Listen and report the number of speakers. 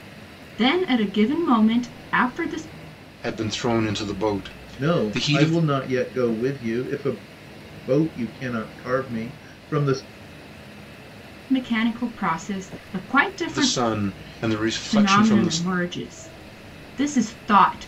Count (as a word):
three